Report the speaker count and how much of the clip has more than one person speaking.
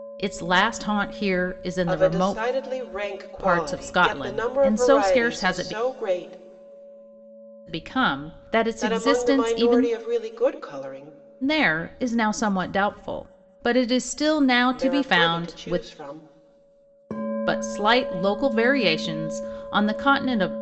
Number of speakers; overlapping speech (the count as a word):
two, about 27%